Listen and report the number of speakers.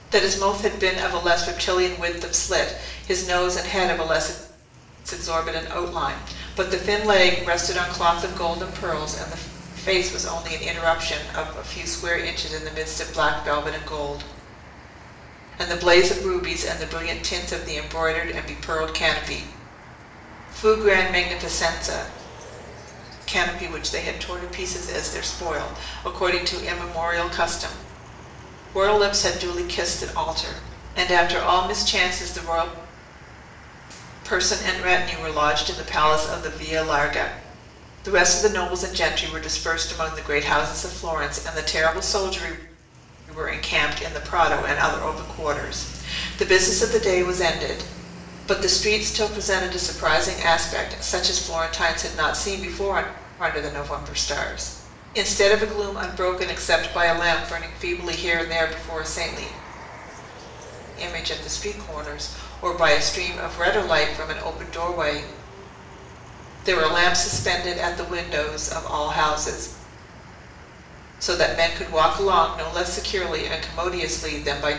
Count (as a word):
one